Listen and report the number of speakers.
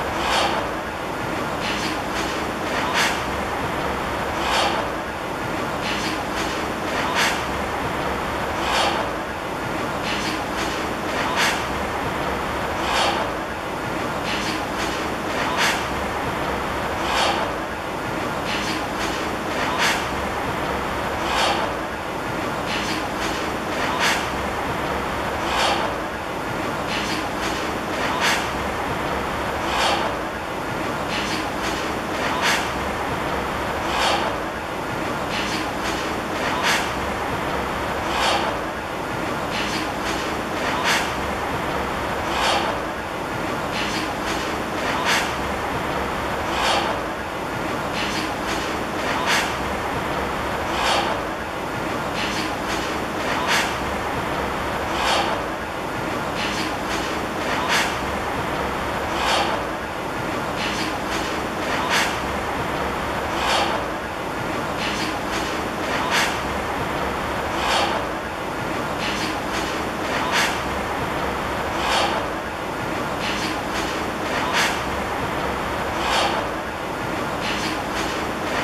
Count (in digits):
0